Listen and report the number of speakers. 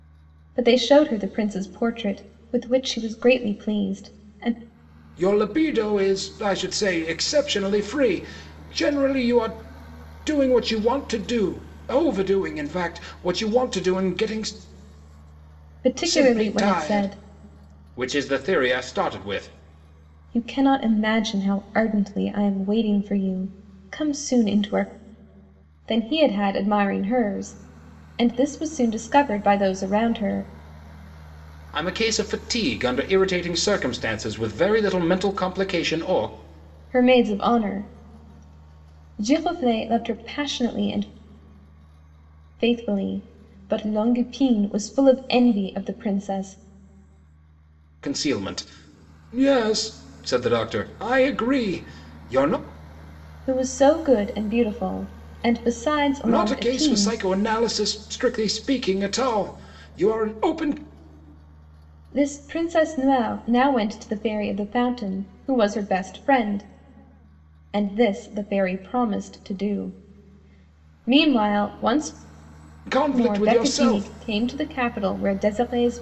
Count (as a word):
two